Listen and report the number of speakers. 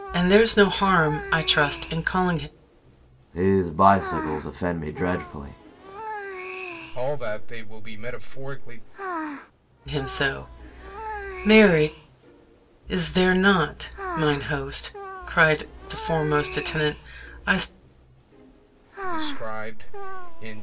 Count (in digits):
3